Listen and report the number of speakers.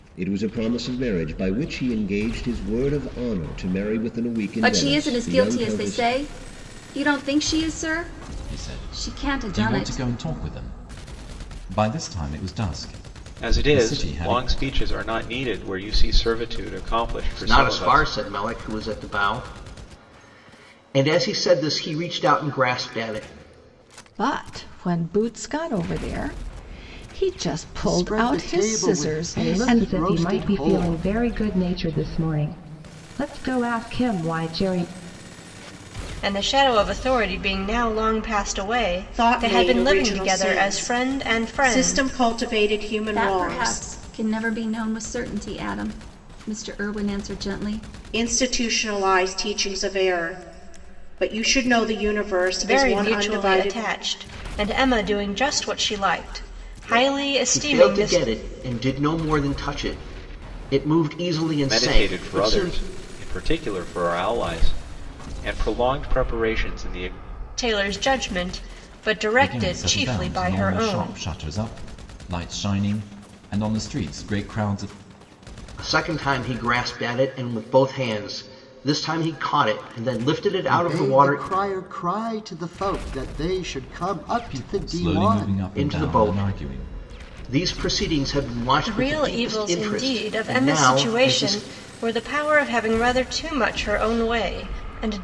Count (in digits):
10